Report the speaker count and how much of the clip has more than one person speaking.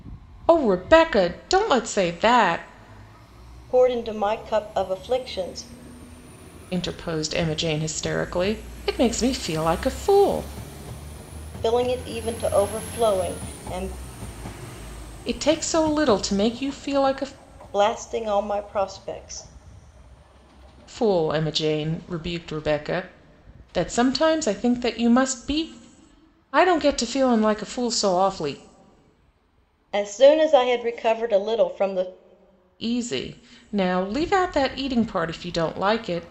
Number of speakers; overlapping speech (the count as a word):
two, no overlap